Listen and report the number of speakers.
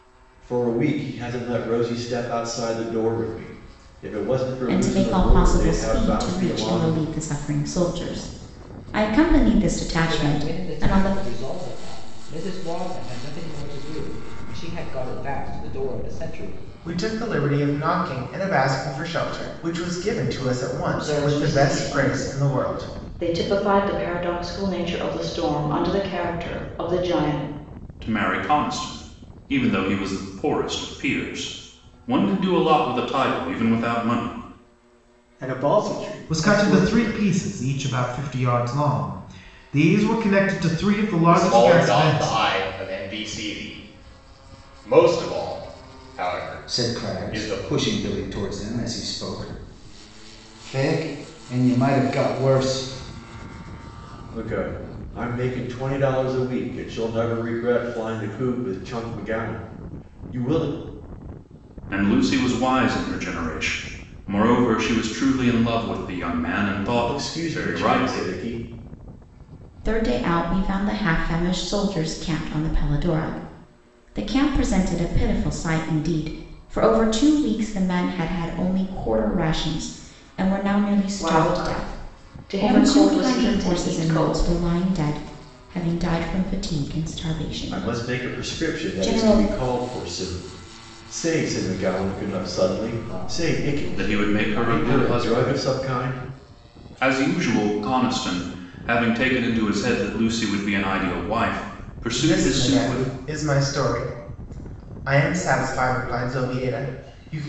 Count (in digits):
10